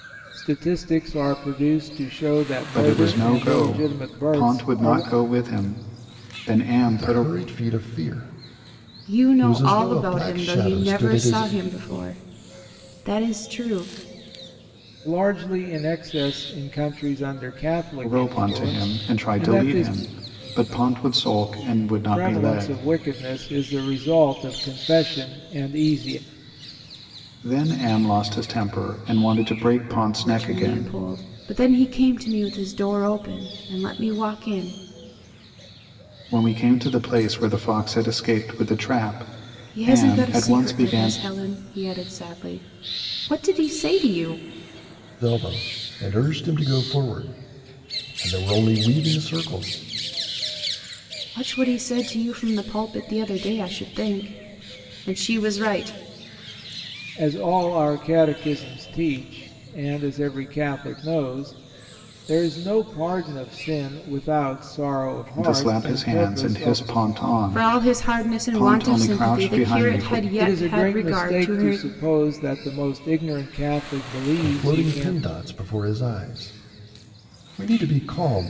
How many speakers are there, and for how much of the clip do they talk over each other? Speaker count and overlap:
4, about 21%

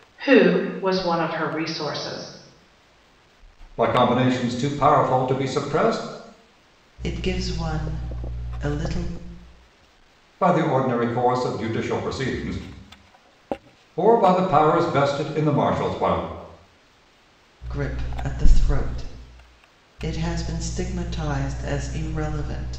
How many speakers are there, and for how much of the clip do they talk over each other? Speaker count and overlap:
3, no overlap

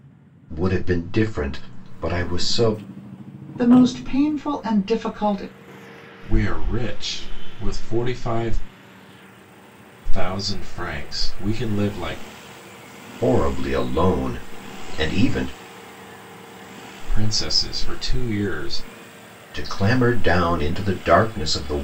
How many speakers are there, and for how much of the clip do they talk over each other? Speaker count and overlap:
3, no overlap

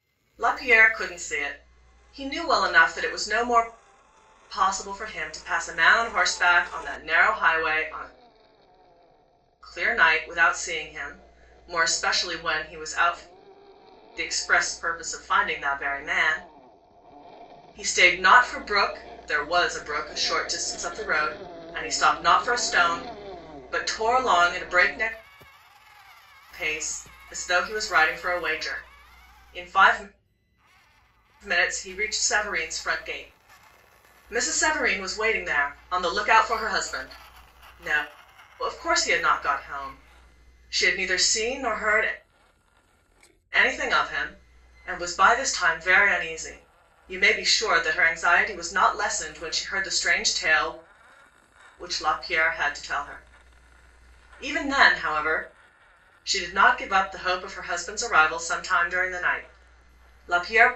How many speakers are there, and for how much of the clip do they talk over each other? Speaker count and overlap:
1, no overlap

